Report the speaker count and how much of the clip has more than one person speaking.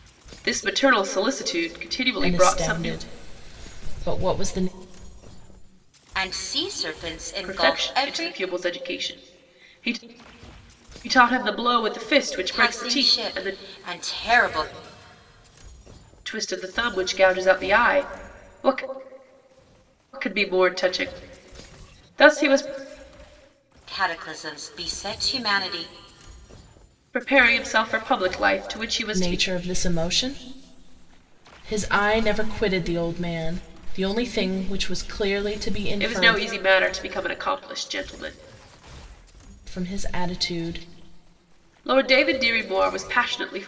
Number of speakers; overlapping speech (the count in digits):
3, about 9%